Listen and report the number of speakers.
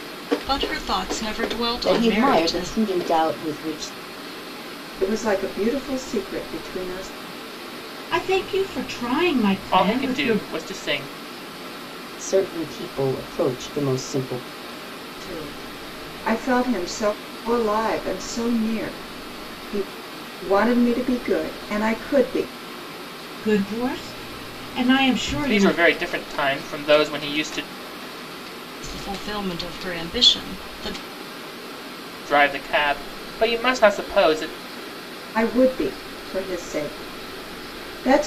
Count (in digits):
5